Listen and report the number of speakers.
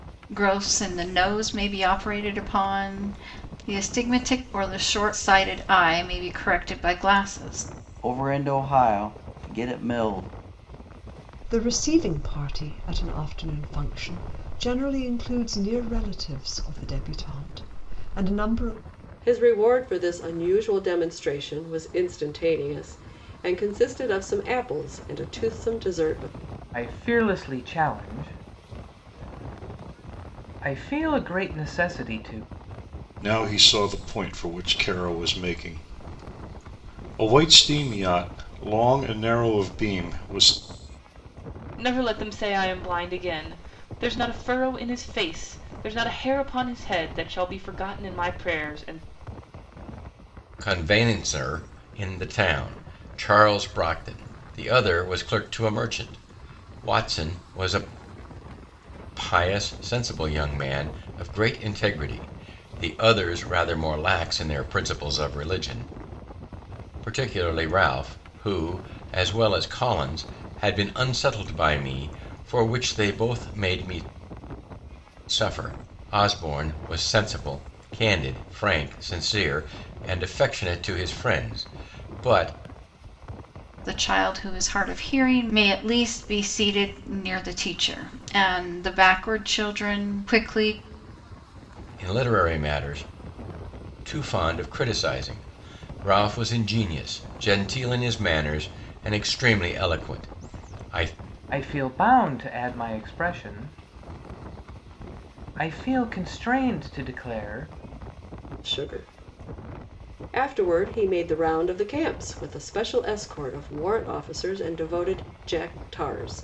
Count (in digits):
8